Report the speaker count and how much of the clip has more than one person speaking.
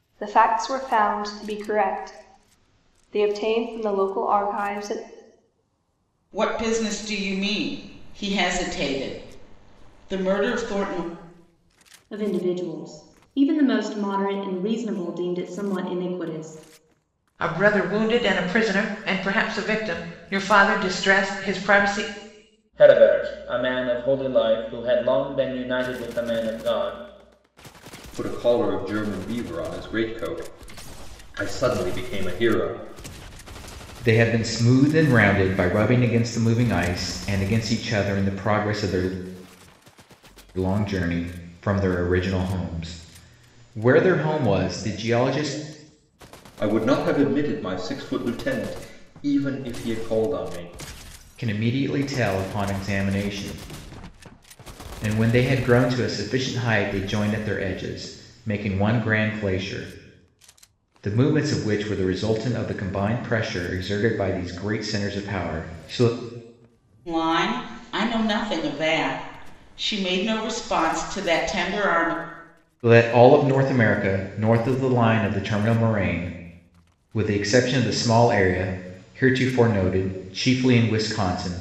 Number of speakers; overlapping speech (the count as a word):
seven, no overlap